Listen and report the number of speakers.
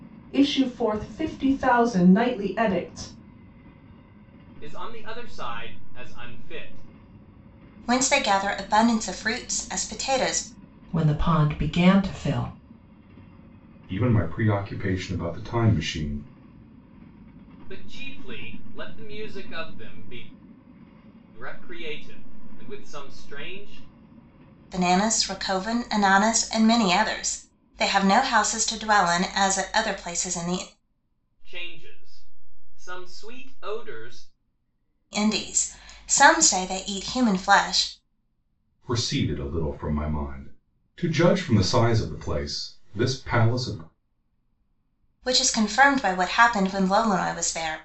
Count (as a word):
five